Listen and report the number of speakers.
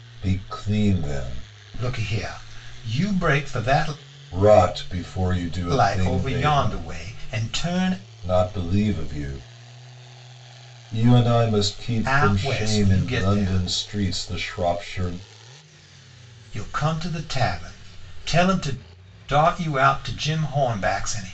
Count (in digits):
2